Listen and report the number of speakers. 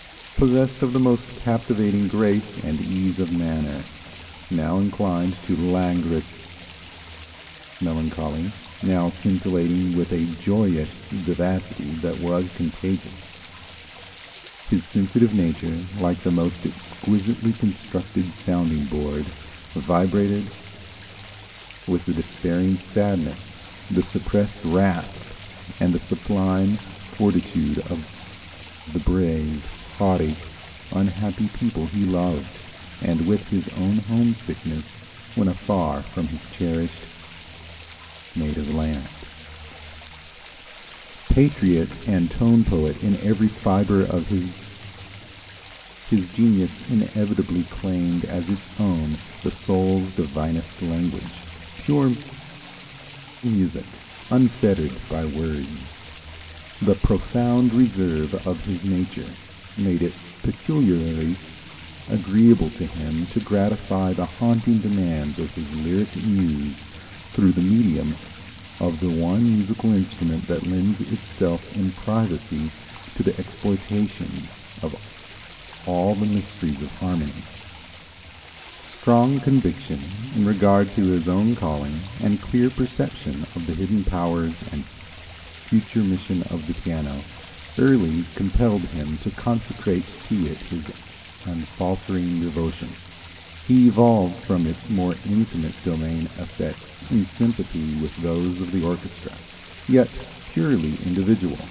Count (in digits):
1